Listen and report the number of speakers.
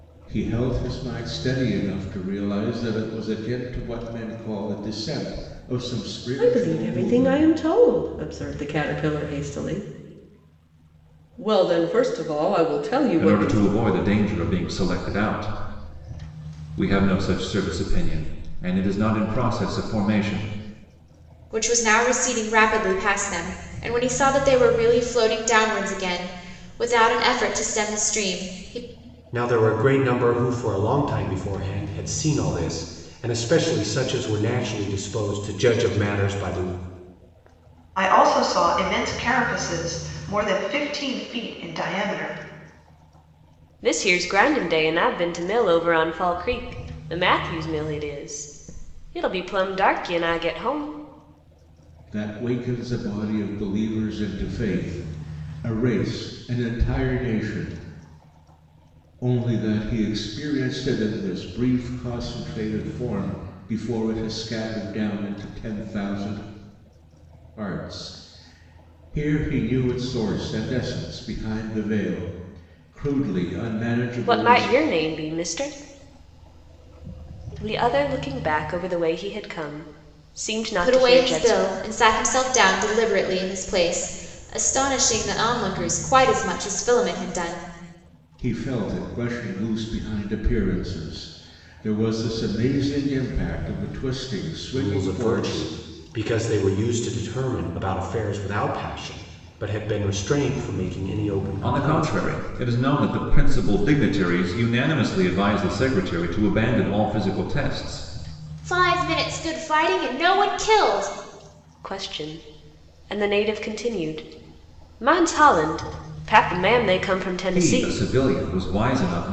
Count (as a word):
seven